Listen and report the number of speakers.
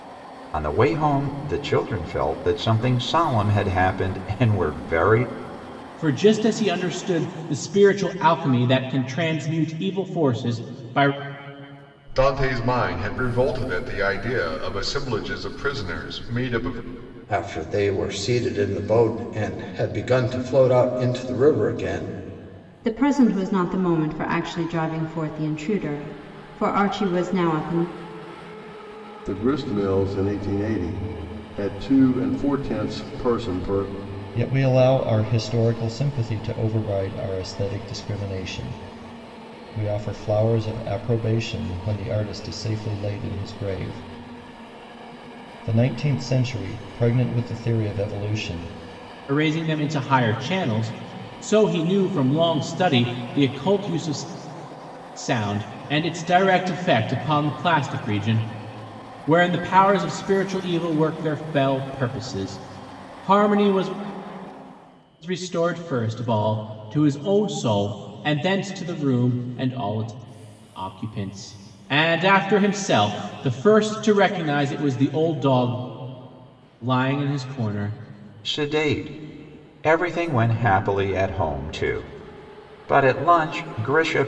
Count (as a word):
seven